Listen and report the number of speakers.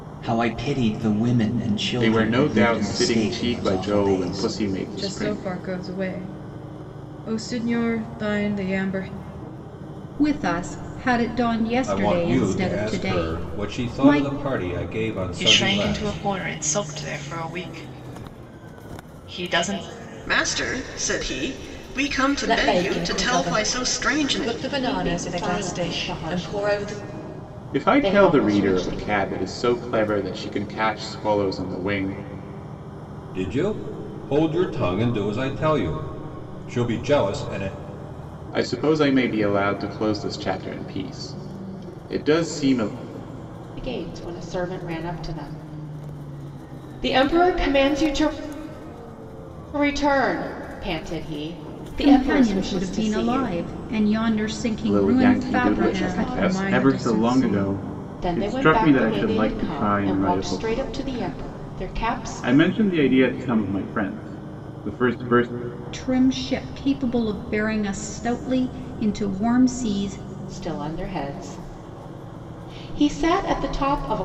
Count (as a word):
nine